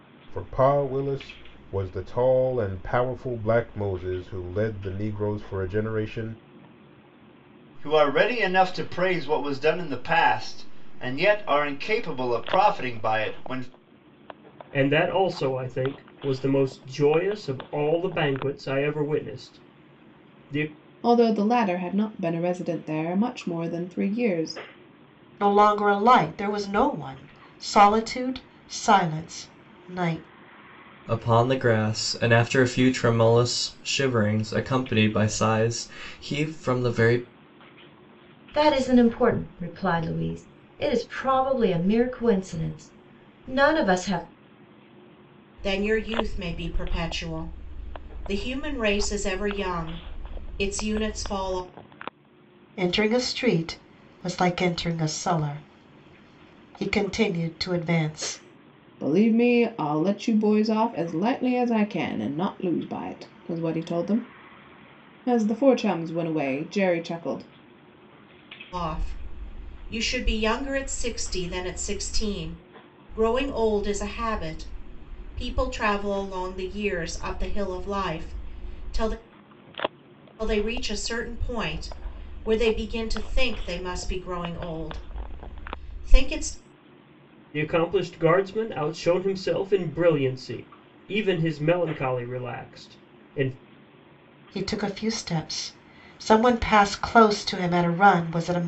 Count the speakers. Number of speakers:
8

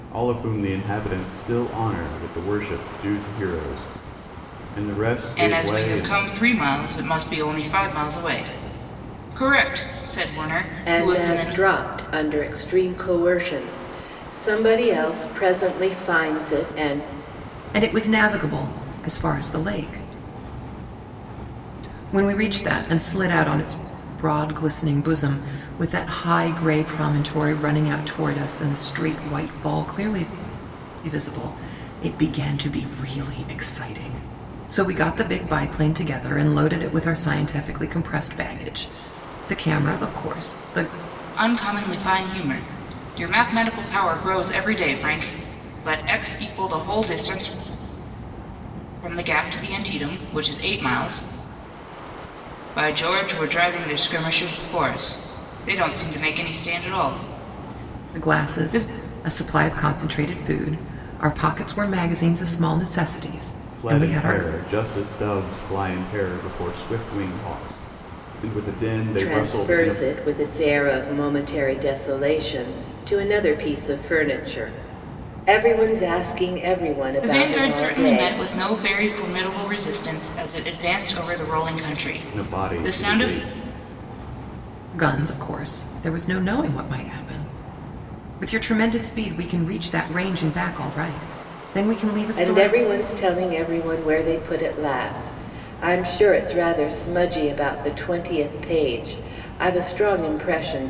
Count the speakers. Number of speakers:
4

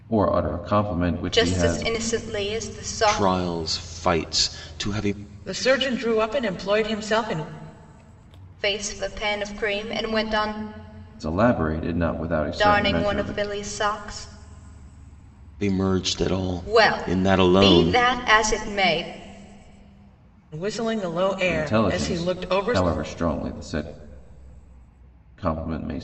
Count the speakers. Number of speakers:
4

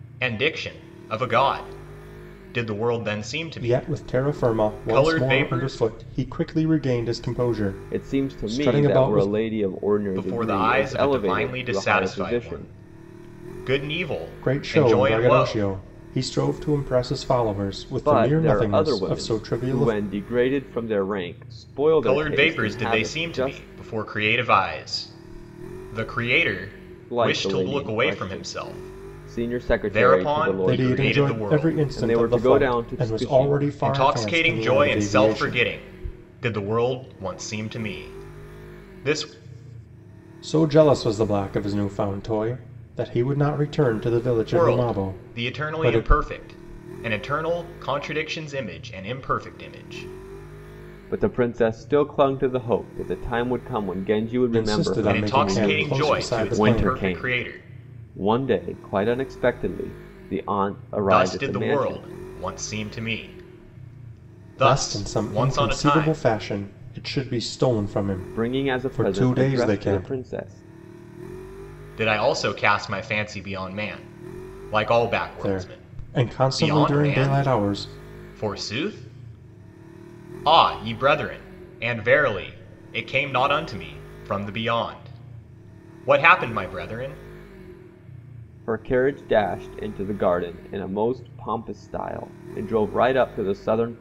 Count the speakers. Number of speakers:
3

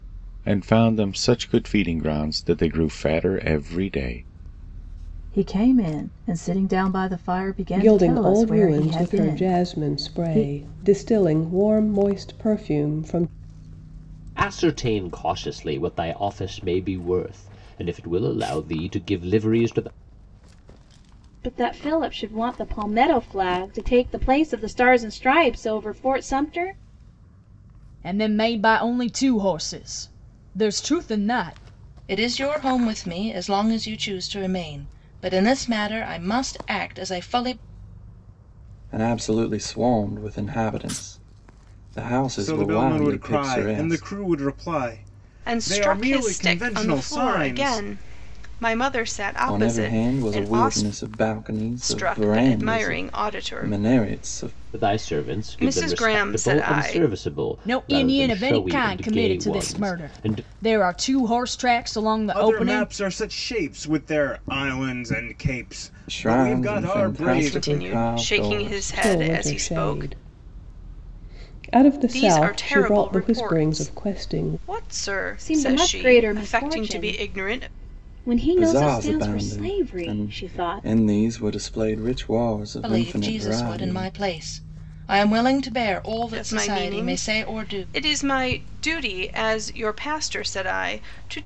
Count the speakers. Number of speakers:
10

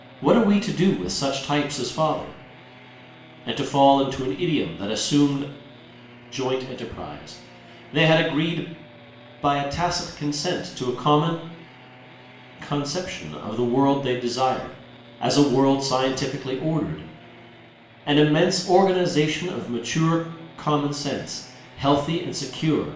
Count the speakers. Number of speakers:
1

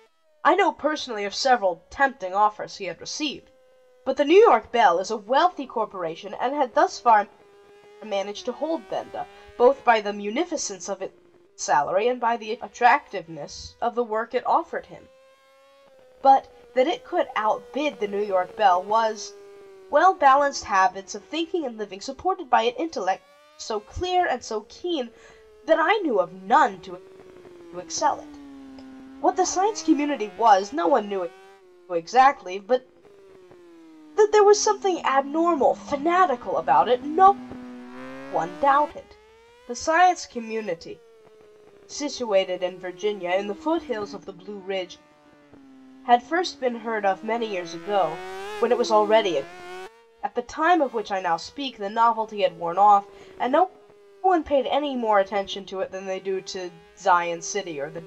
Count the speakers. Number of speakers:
1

